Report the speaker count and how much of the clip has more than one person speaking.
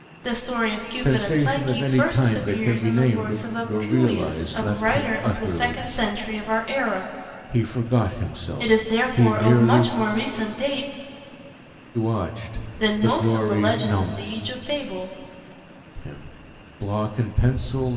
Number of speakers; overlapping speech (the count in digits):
2, about 42%